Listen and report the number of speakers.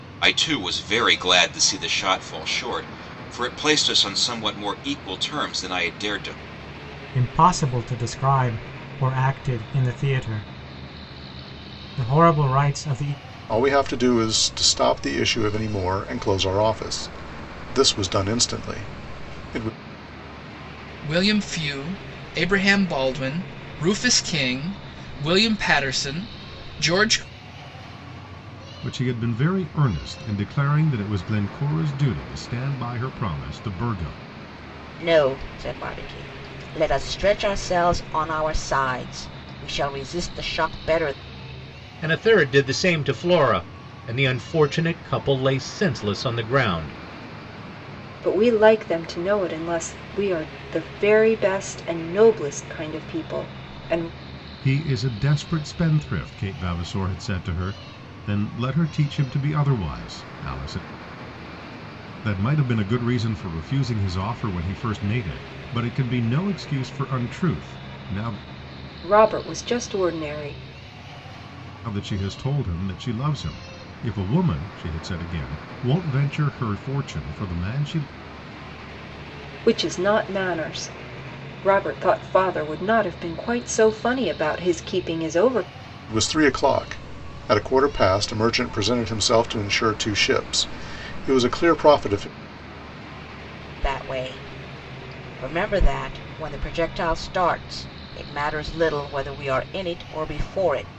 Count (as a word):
eight